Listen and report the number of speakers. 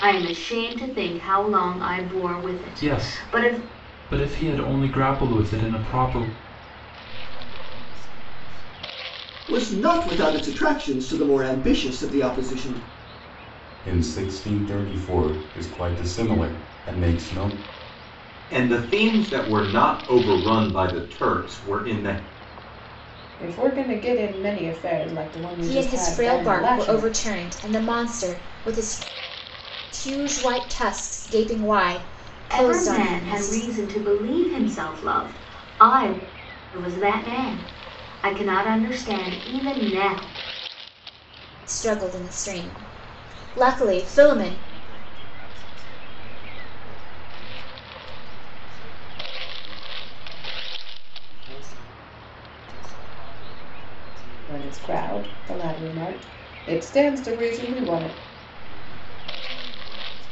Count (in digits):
8